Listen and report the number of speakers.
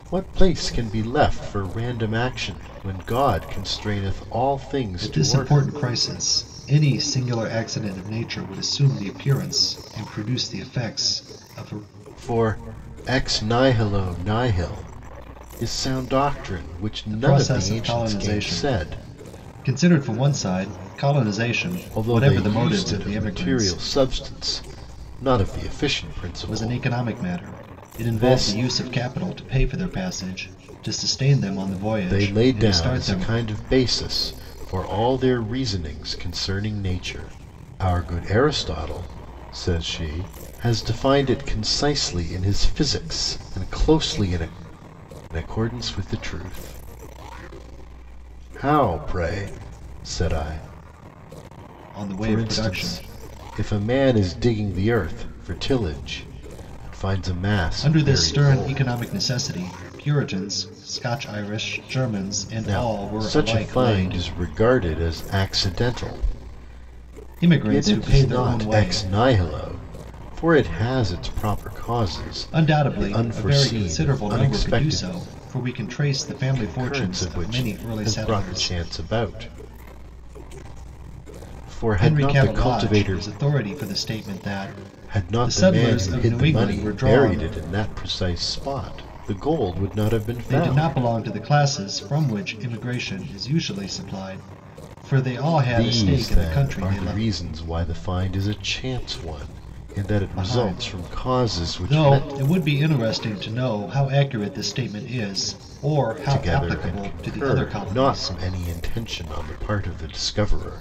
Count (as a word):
two